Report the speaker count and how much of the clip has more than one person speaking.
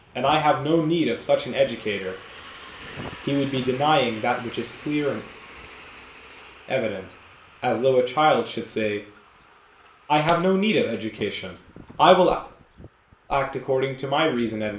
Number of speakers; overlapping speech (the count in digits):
1, no overlap